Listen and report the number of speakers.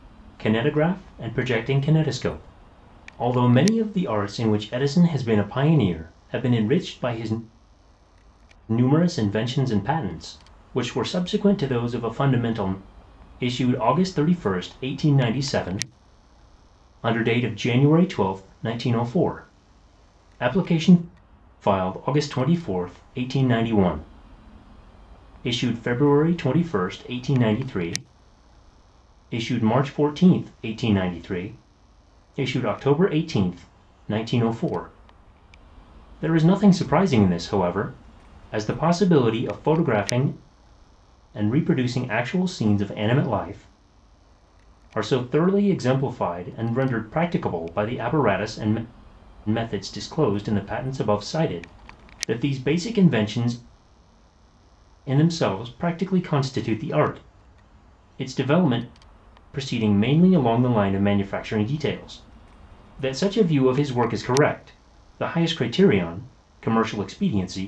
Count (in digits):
1